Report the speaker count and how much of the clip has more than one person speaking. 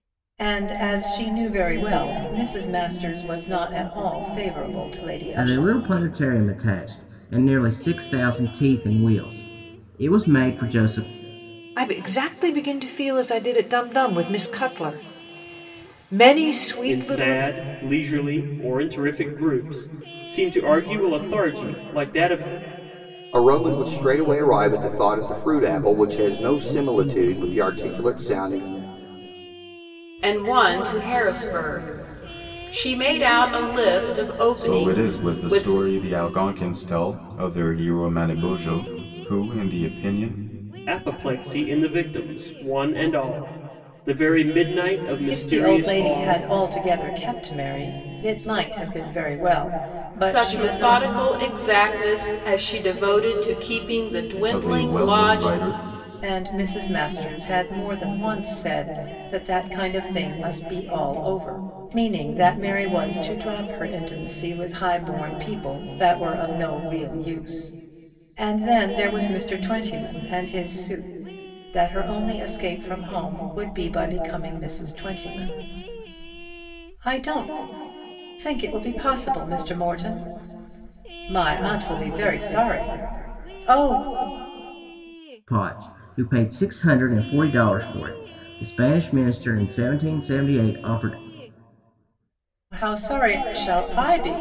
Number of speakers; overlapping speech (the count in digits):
7, about 6%